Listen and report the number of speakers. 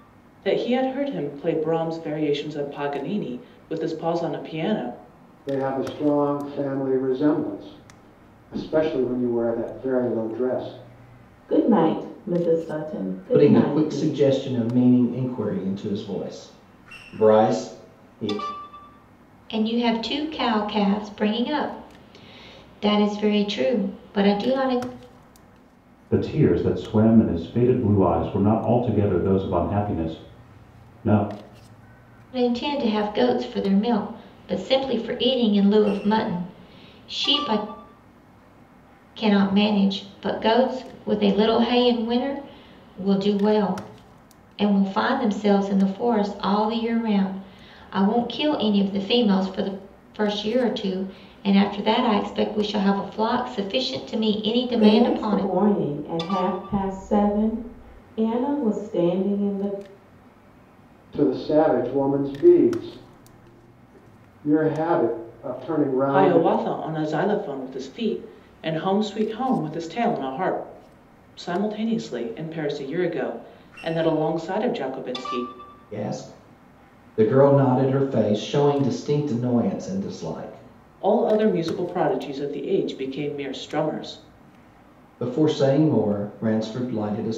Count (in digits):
6